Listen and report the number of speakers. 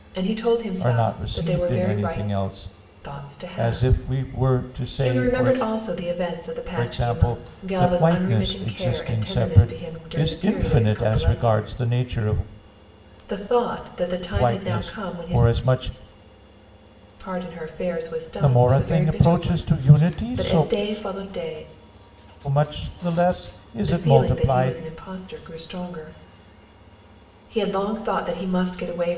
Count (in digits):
2